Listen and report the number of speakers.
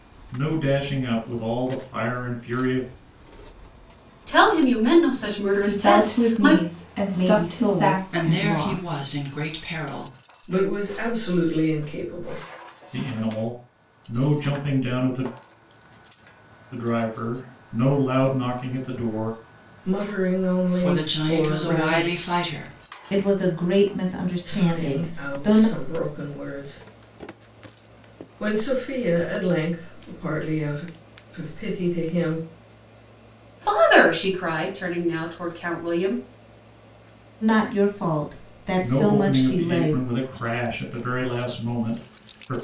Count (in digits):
6